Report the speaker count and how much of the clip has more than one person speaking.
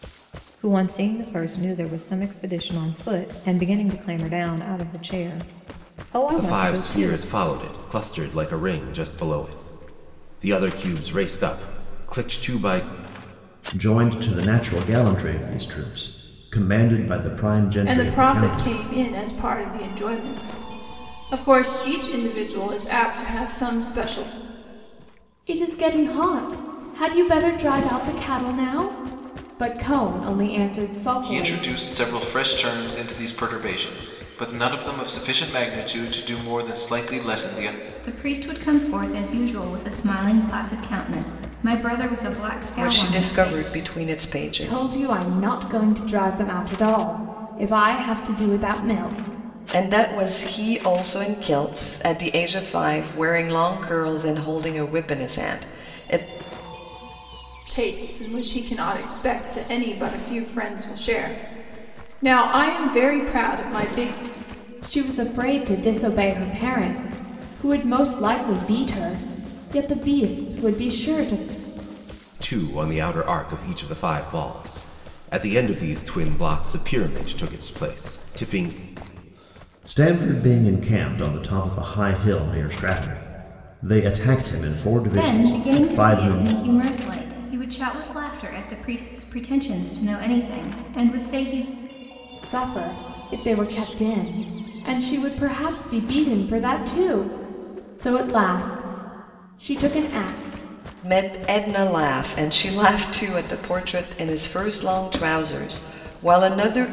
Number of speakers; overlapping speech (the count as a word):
eight, about 5%